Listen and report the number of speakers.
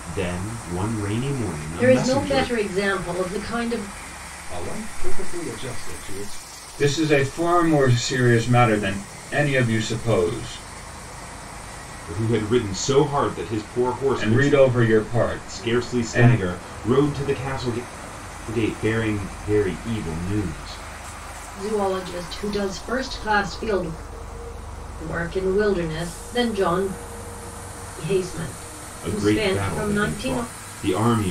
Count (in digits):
4